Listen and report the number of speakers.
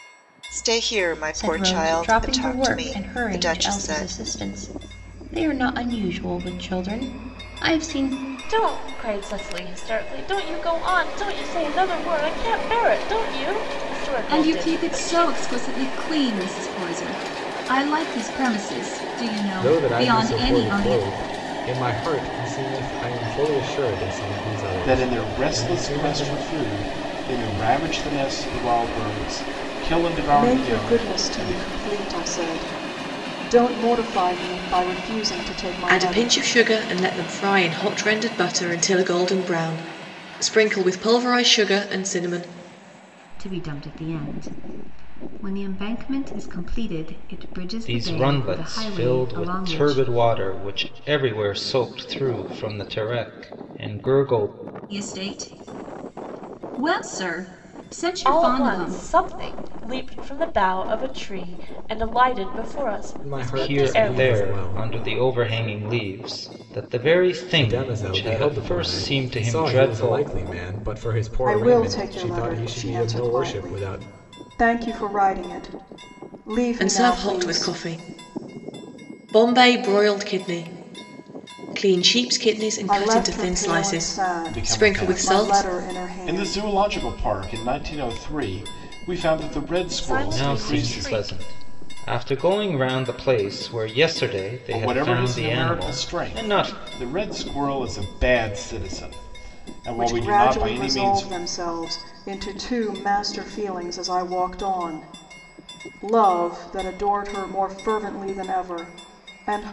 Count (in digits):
10